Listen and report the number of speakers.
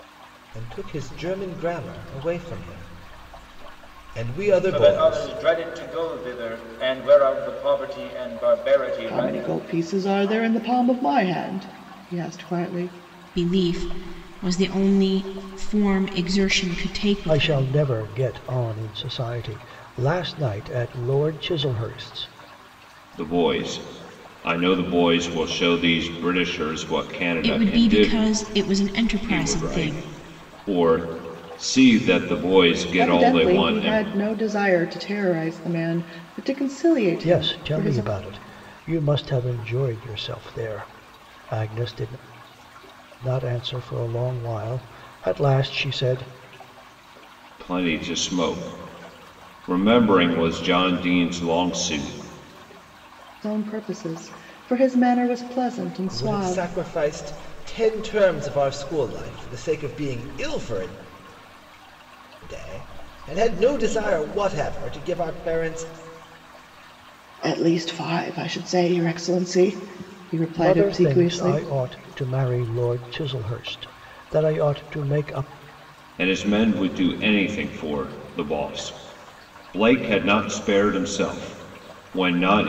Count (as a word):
six